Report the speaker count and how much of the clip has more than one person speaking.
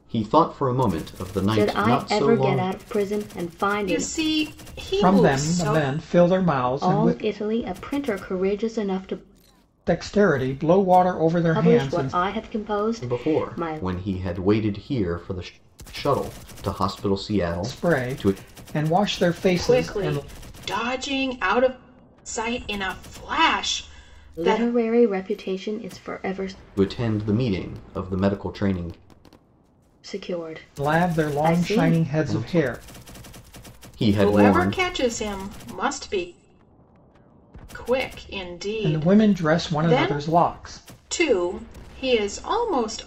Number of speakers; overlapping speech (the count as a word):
four, about 24%